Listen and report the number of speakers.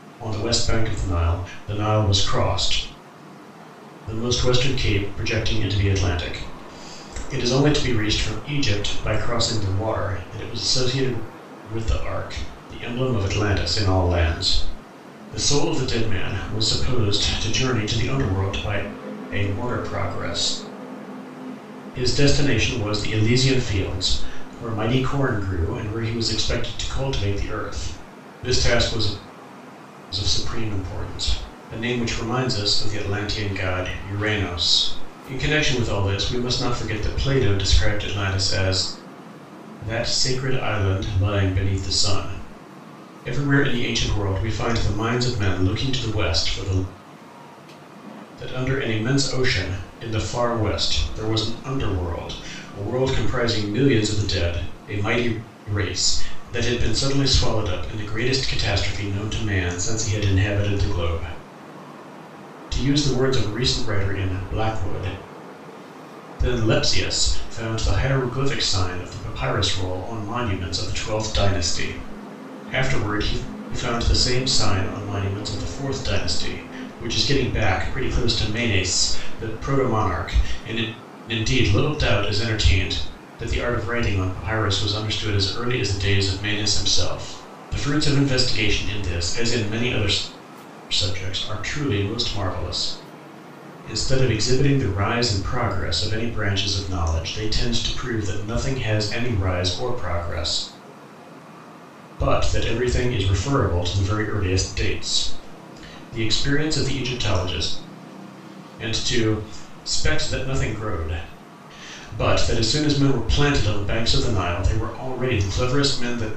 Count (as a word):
one